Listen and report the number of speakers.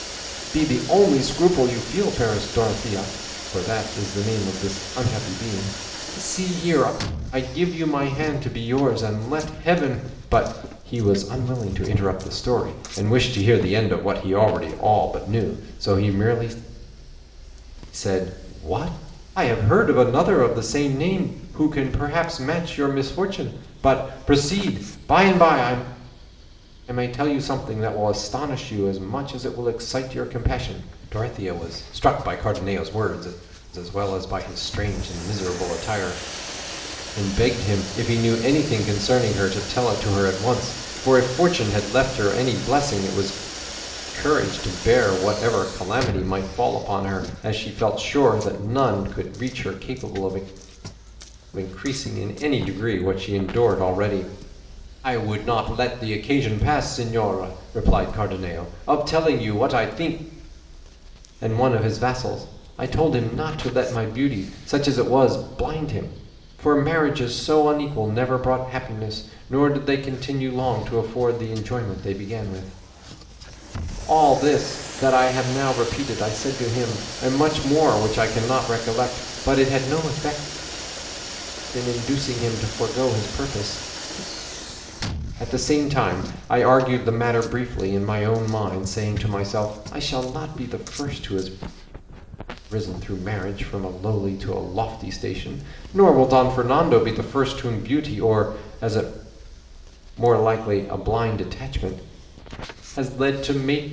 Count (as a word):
one